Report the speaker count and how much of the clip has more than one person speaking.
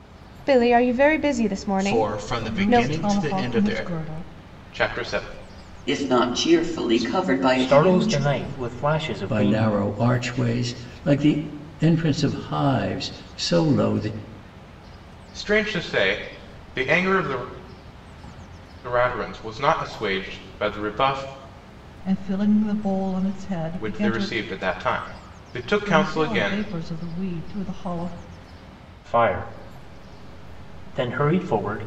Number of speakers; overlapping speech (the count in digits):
7, about 18%